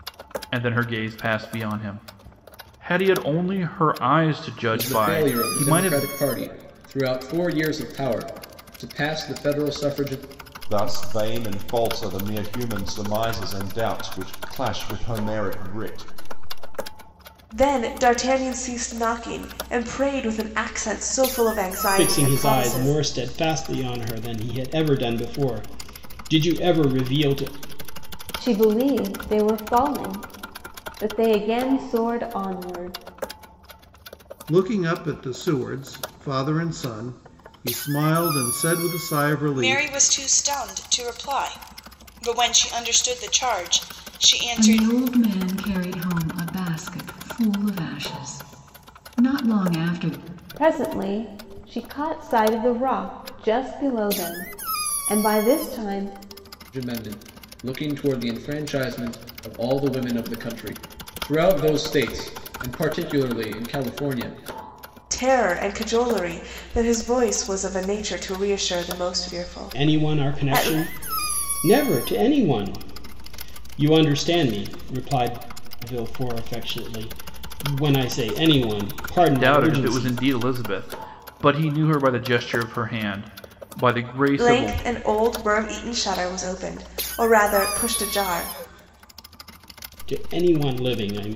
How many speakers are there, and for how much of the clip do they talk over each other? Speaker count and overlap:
9, about 6%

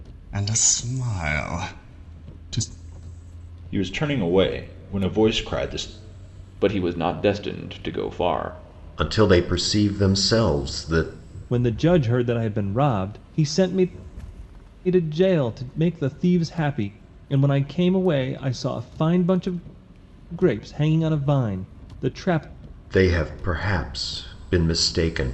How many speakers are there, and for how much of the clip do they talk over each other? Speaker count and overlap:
5, no overlap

